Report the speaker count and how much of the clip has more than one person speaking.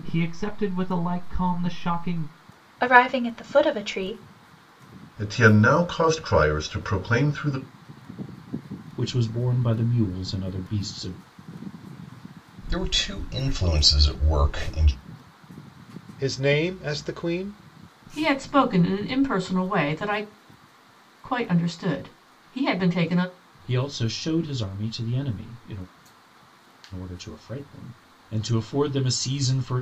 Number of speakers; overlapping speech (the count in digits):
7, no overlap